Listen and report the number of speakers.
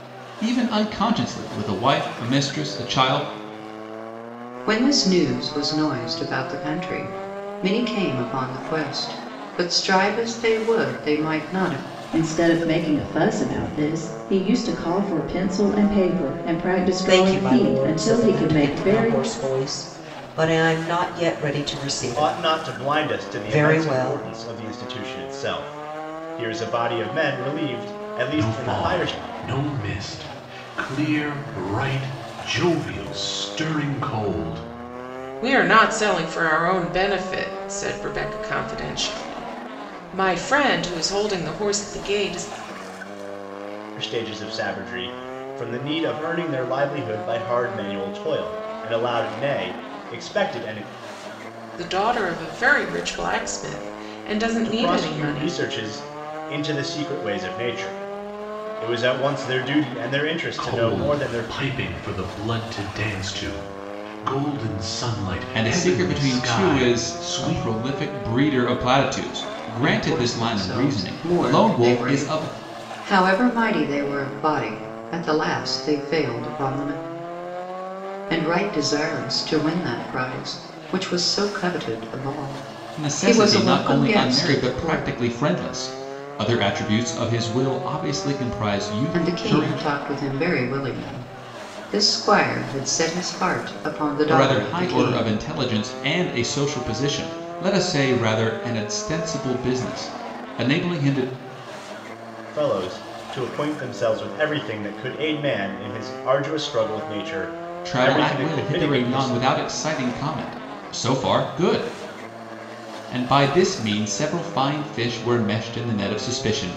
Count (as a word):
seven